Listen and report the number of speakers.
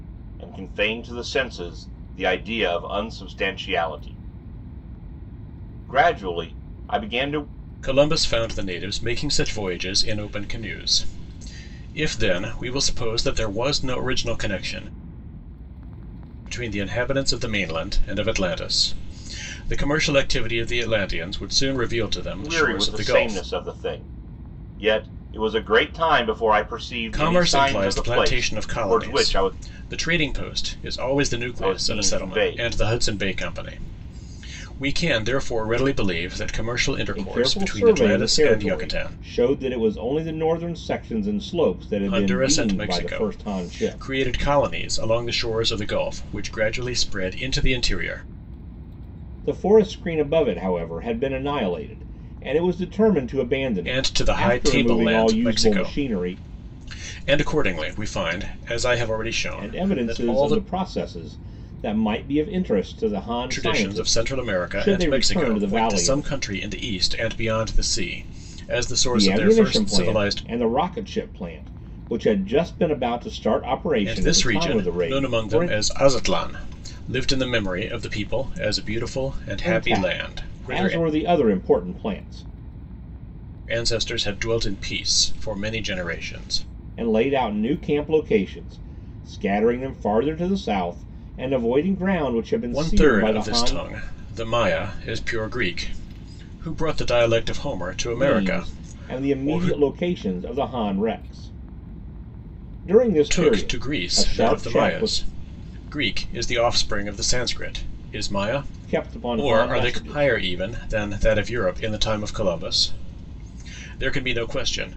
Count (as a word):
two